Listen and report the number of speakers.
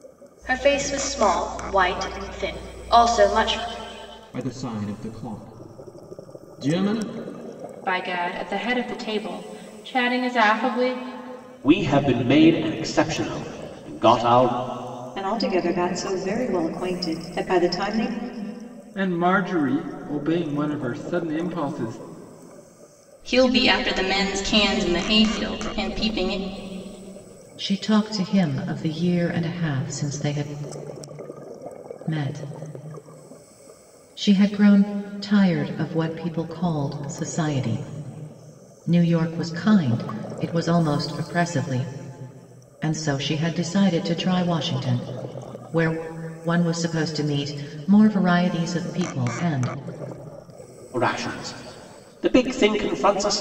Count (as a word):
eight